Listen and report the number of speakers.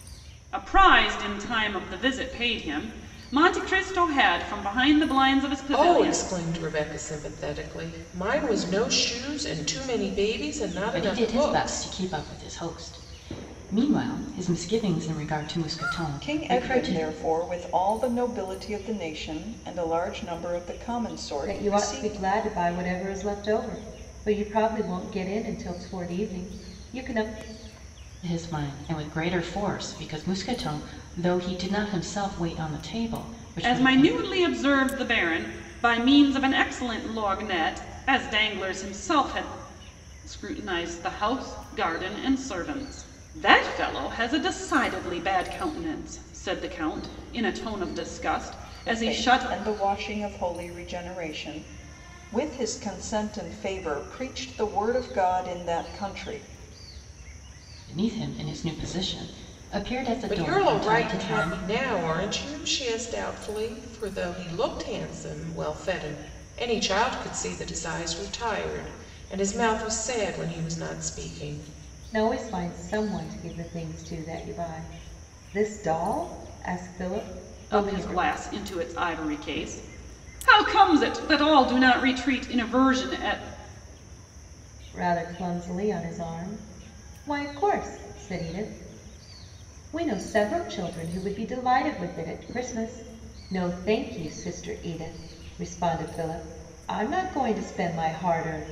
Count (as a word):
five